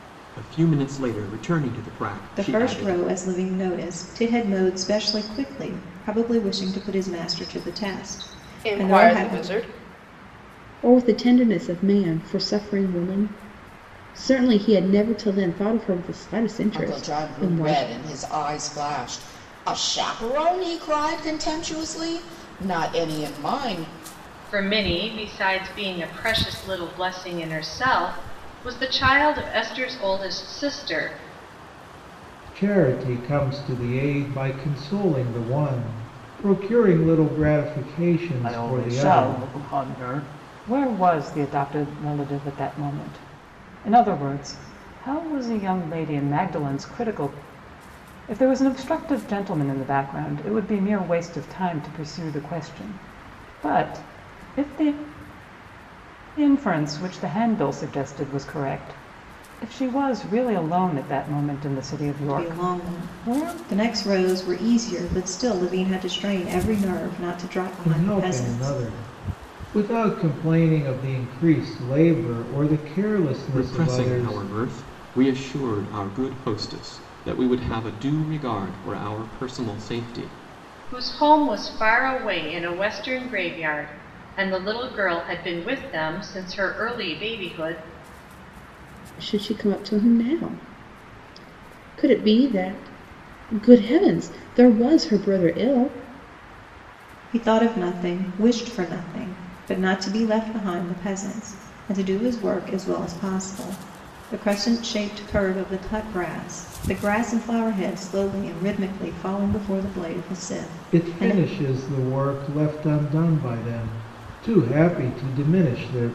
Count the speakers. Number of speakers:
eight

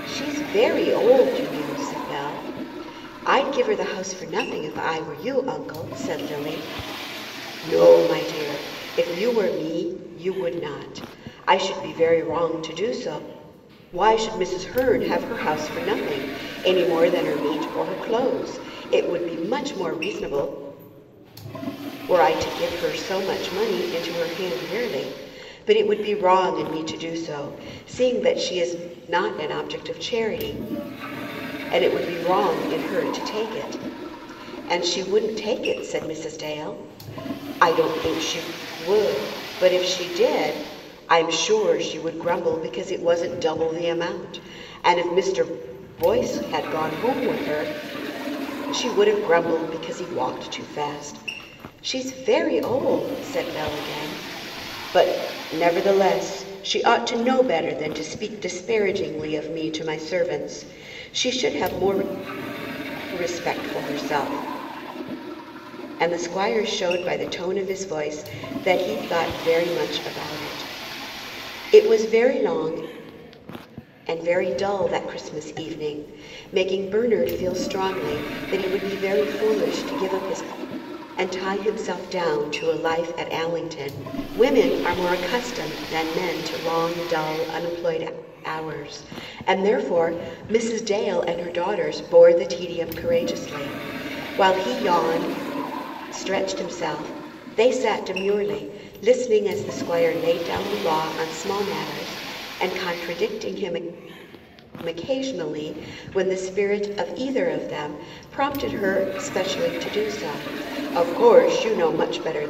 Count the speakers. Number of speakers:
one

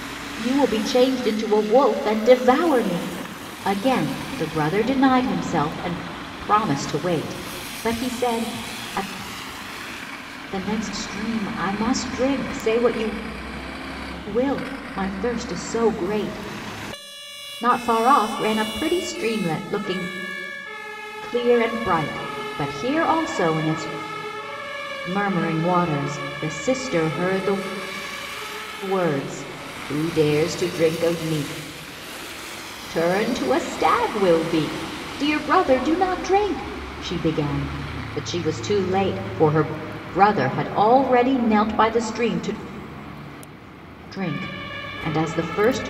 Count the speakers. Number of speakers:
one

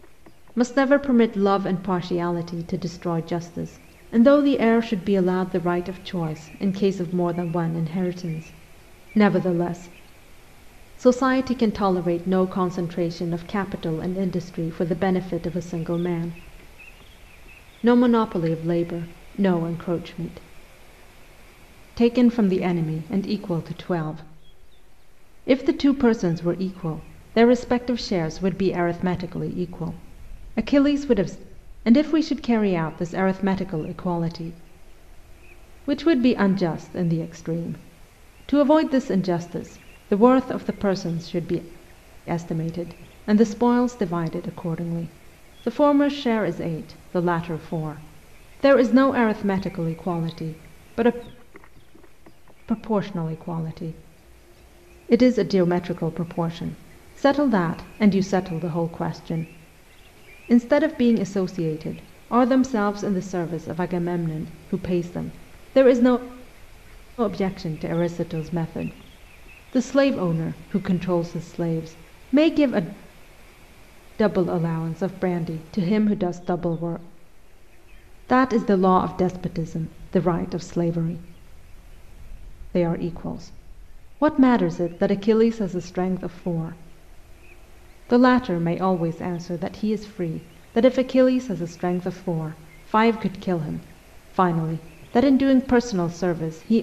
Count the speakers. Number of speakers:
one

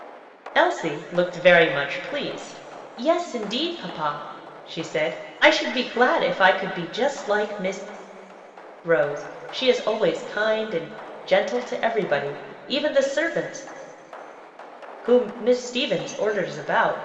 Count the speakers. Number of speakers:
one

